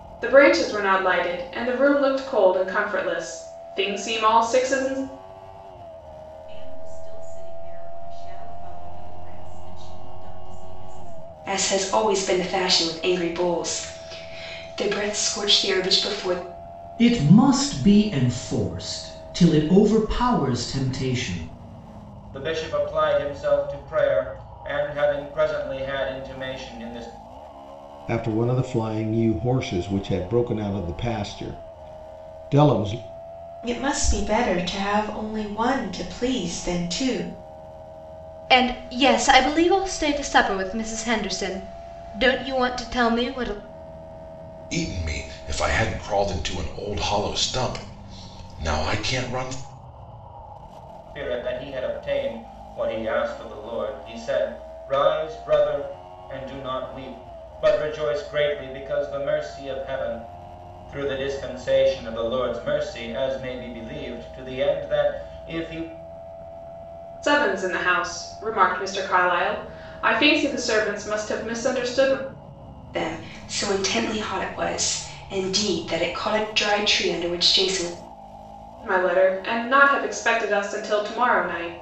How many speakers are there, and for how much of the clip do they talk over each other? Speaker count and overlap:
9, no overlap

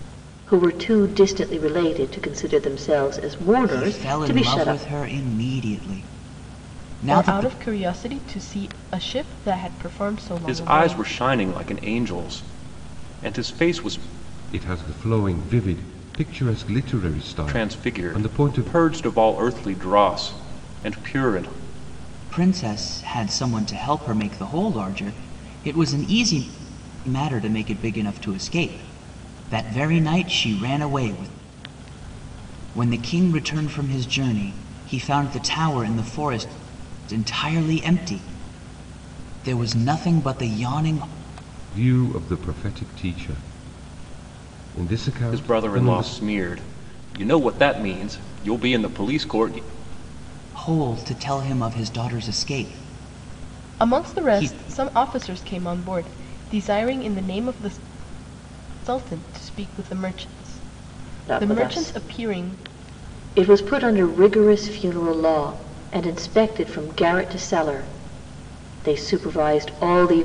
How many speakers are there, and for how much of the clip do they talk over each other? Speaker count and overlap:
5, about 10%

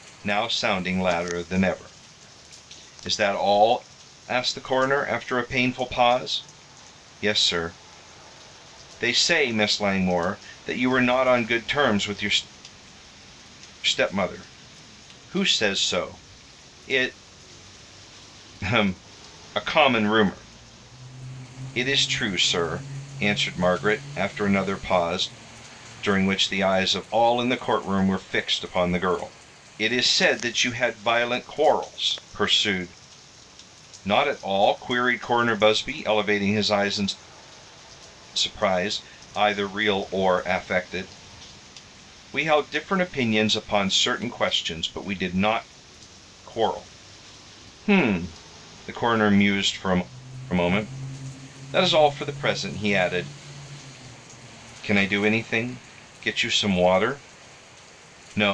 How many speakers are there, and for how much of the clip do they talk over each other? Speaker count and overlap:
1, no overlap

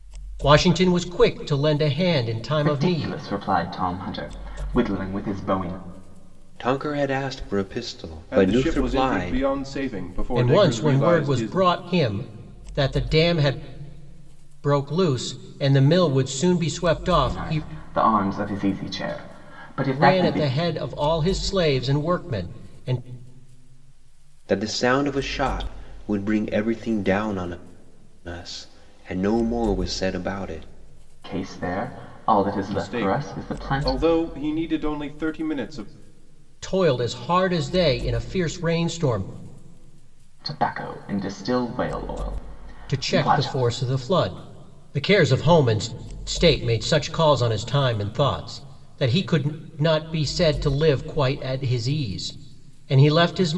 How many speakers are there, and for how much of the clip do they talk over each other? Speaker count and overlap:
4, about 12%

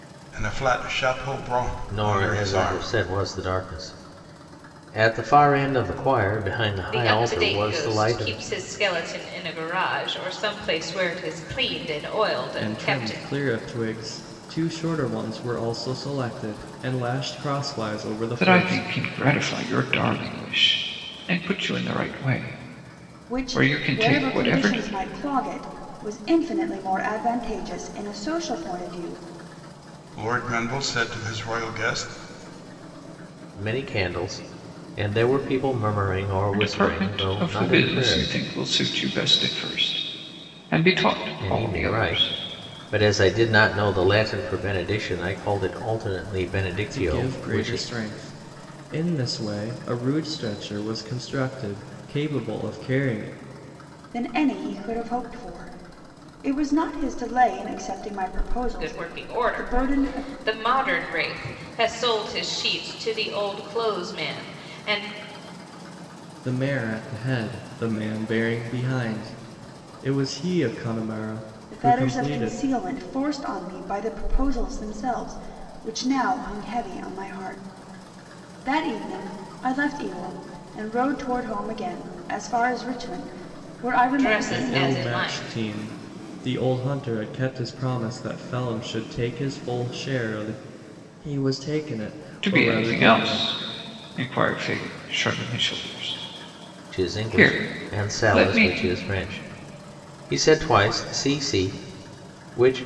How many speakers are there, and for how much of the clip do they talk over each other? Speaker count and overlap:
6, about 16%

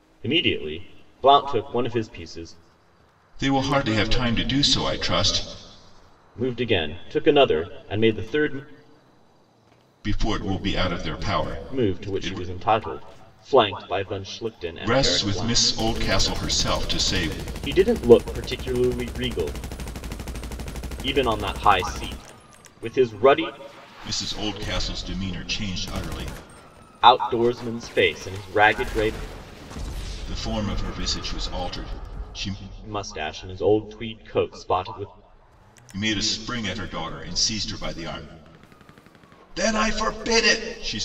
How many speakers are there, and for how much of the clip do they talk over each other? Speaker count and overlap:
2, about 4%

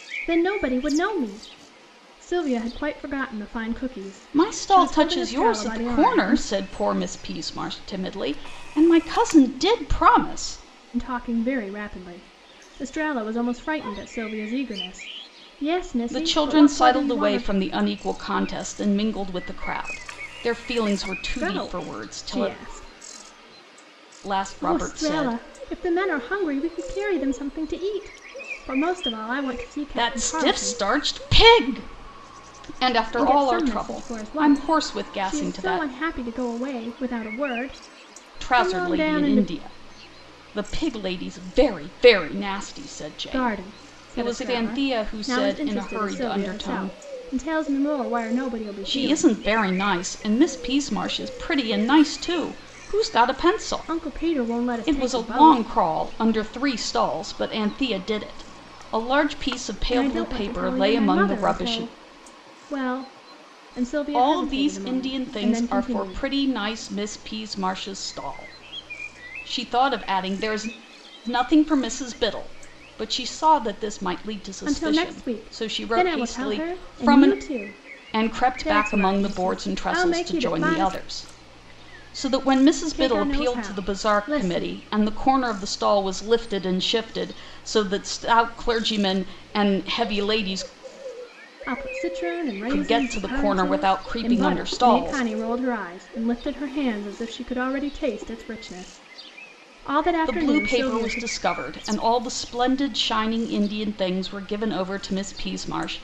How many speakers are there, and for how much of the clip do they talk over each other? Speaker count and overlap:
2, about 30%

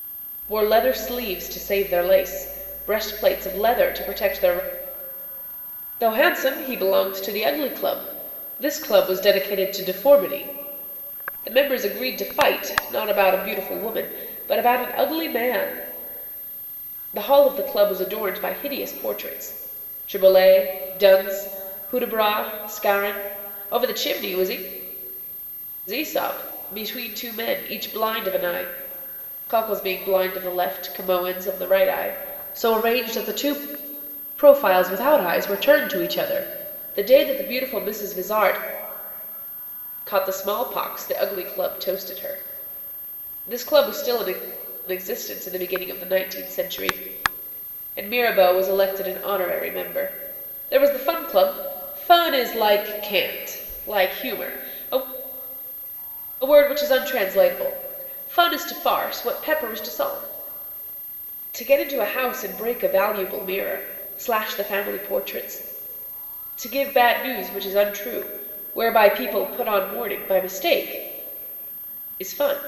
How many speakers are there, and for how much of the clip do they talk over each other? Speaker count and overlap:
1, no overlap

